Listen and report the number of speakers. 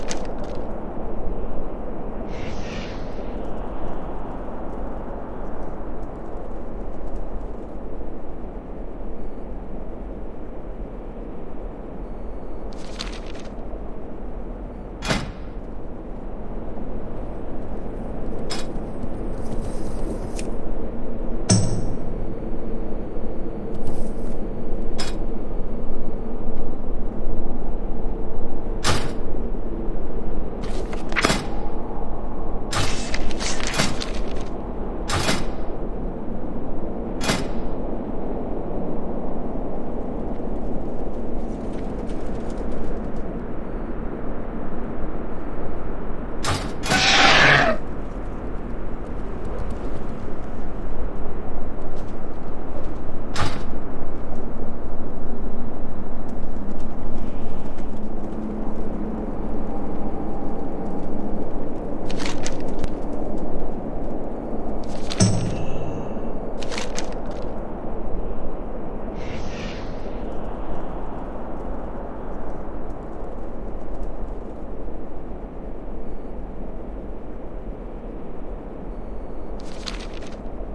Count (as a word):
zero